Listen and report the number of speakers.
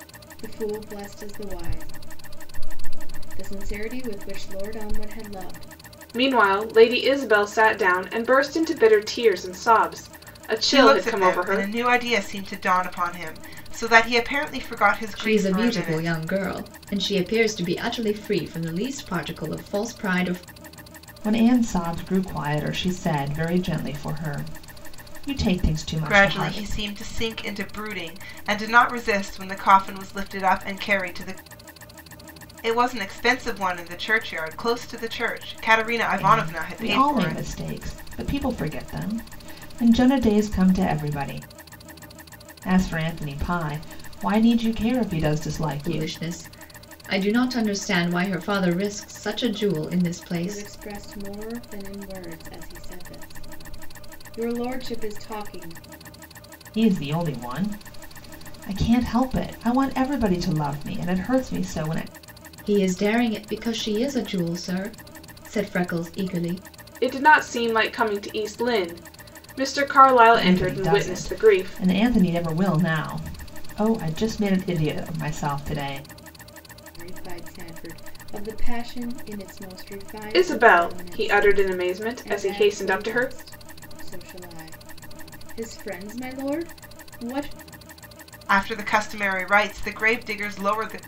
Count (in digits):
5